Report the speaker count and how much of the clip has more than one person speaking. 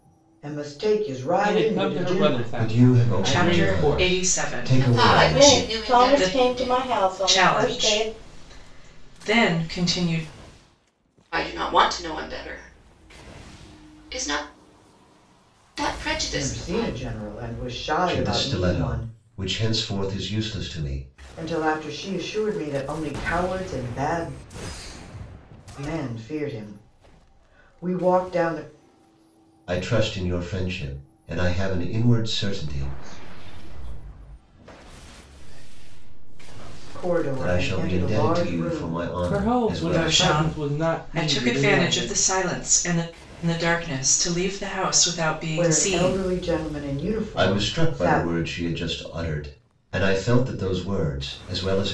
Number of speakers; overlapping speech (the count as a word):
seven, about 31%